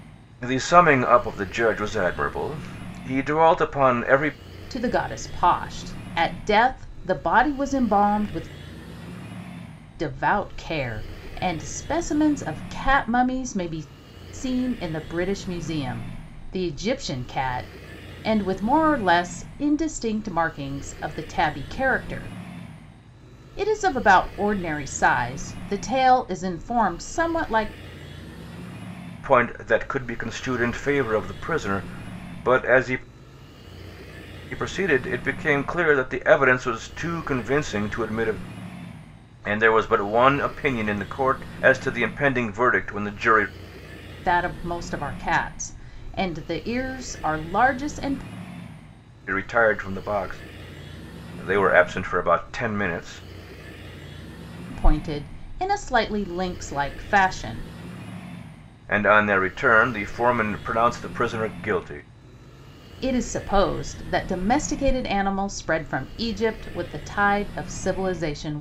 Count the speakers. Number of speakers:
2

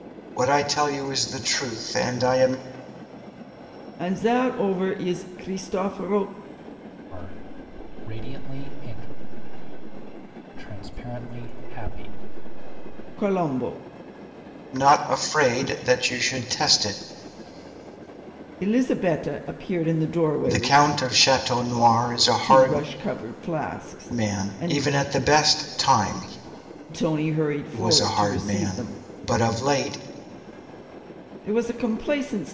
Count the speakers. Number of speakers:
3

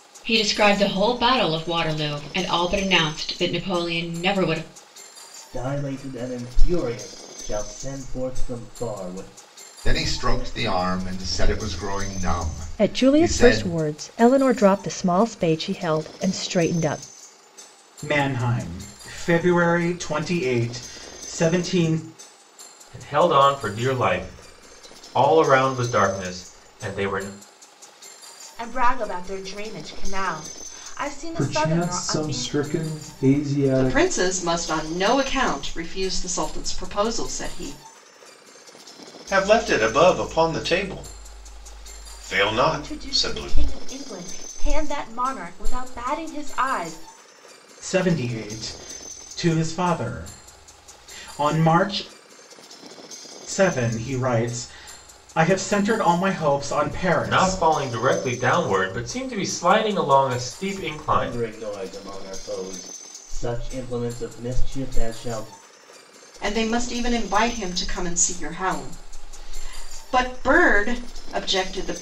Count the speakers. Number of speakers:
10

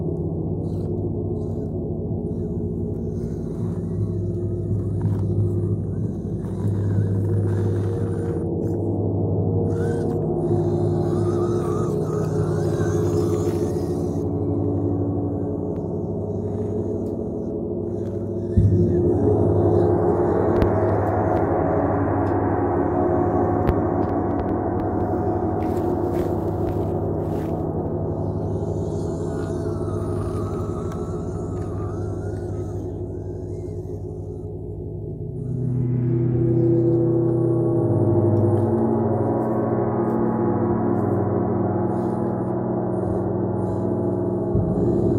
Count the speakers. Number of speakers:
0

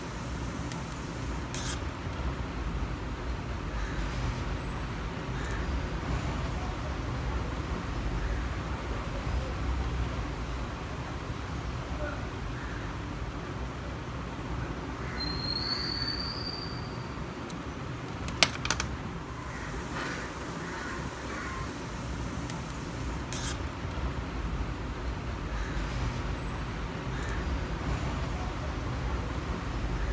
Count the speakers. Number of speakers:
0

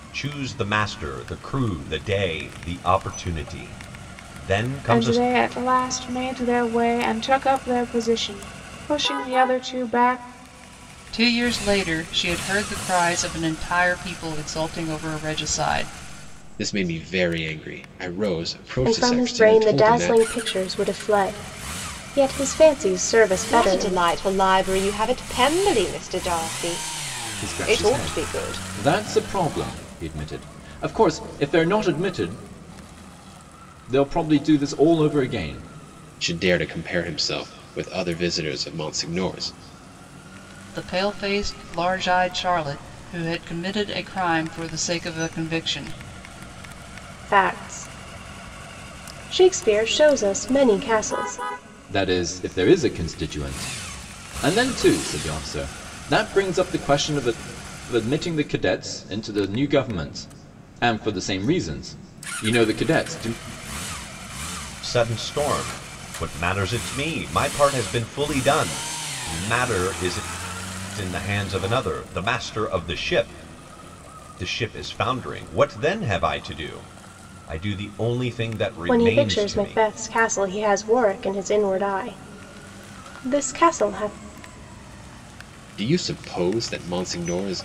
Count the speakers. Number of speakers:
7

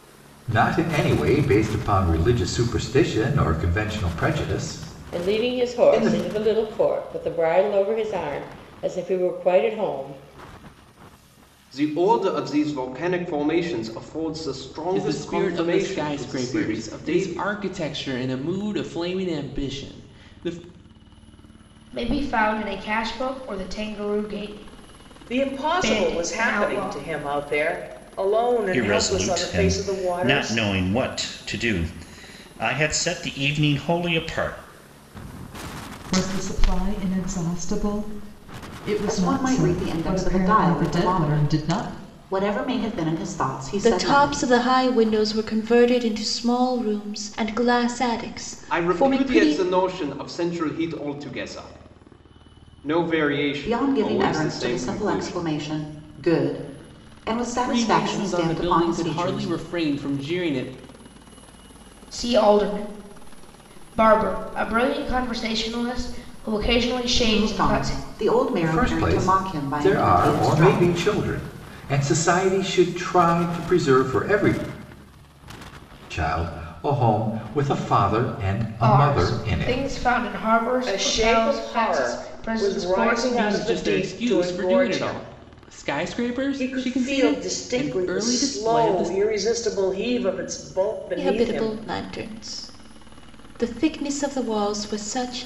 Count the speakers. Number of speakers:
10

